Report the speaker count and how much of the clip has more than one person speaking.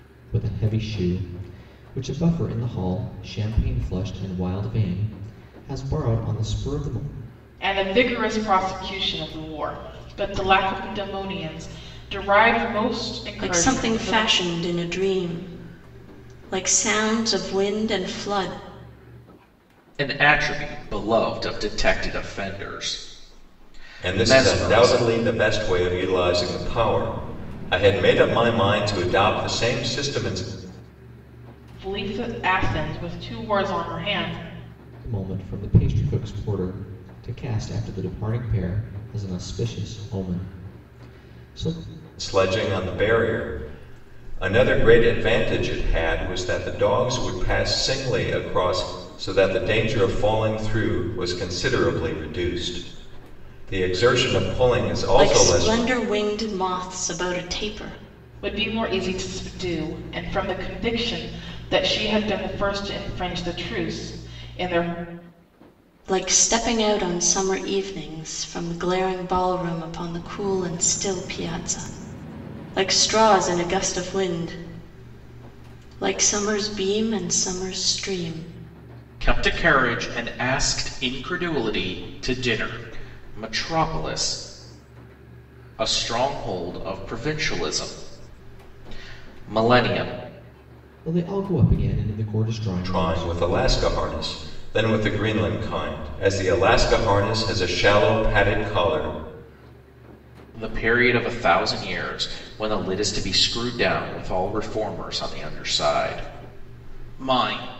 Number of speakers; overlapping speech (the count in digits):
5, about 3%